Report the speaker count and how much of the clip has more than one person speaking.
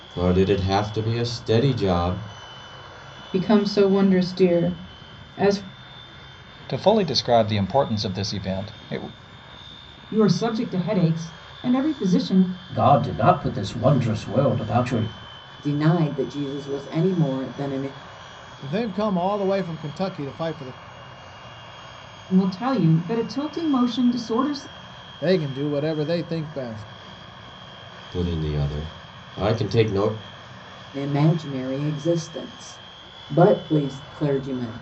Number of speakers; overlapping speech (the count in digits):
7, no overlap